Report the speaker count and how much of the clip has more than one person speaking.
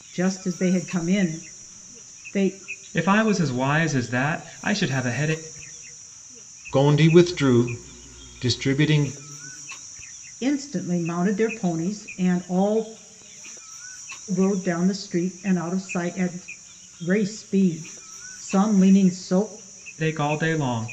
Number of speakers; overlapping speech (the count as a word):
three, no overlap